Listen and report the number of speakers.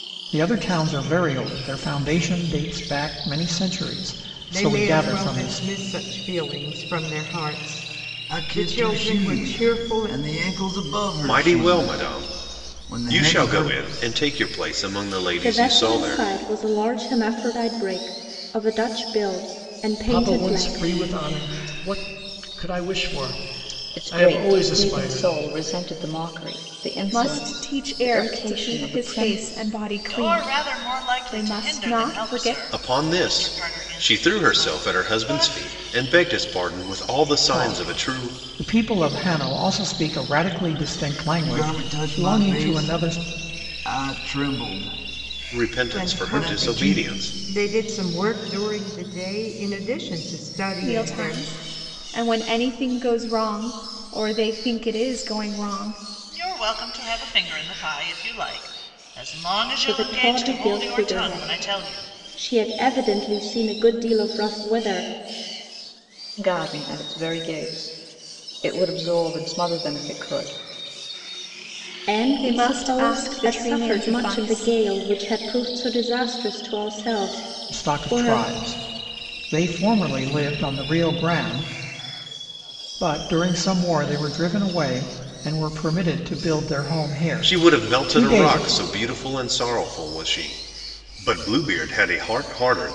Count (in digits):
9